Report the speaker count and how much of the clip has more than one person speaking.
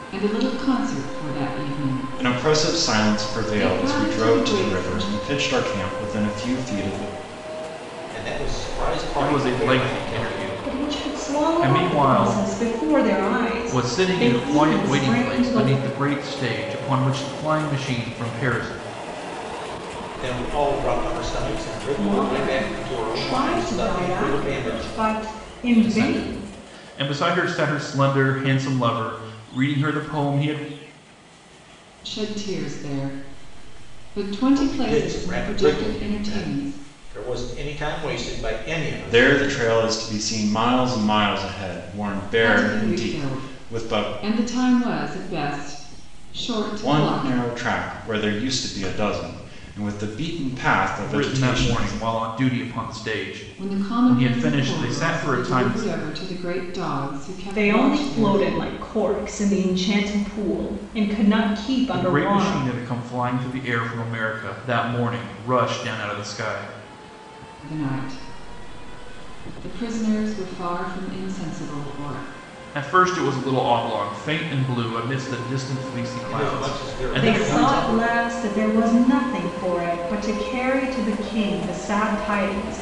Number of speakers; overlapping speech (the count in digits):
5, about 29%